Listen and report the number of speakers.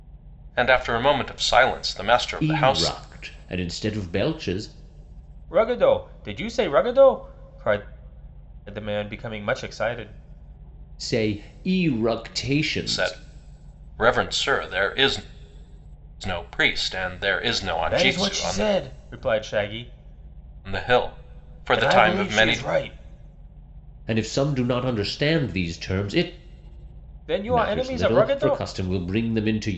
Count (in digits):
3